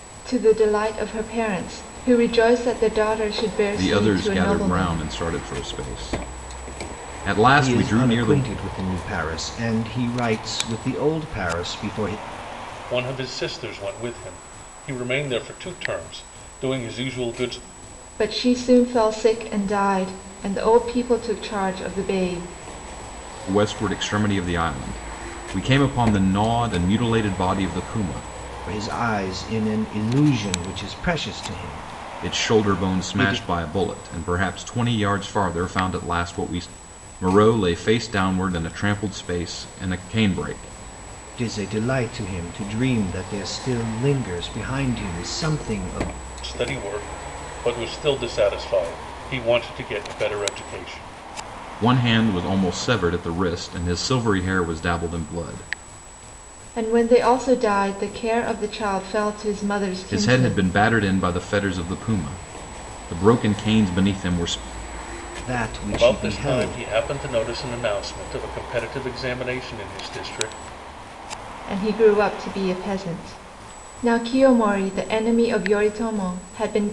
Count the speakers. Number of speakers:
4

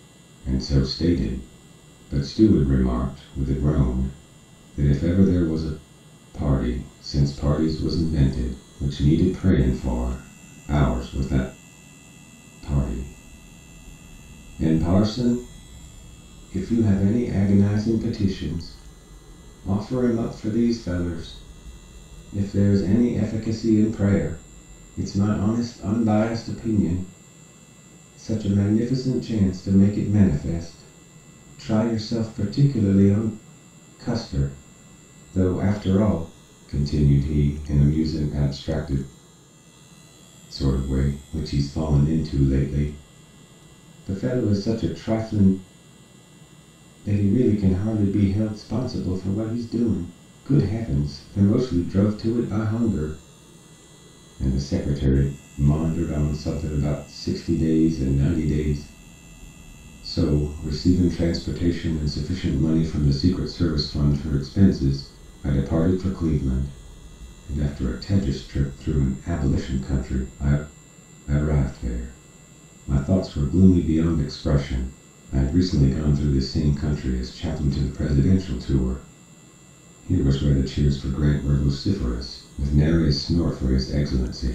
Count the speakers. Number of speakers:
1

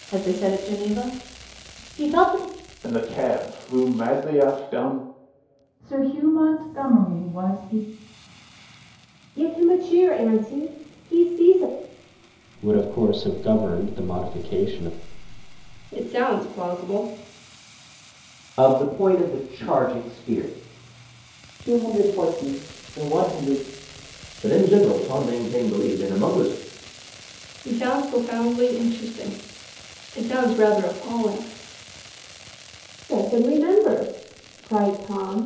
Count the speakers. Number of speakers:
9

